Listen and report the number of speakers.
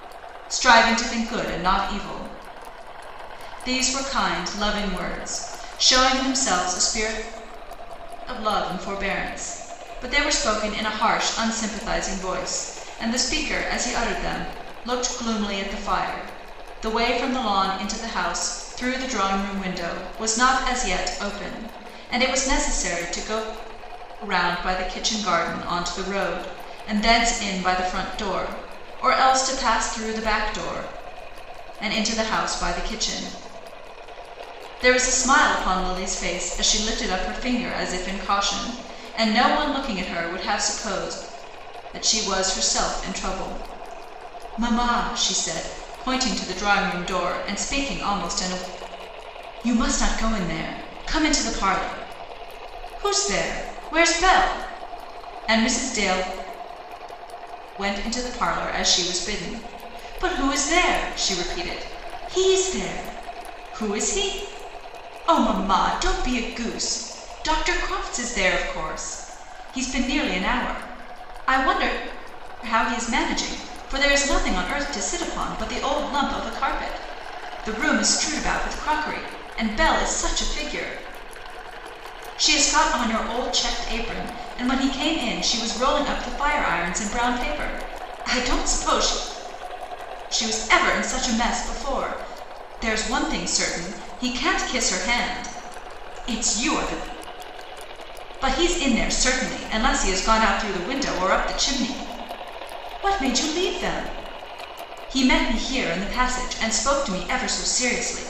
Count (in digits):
1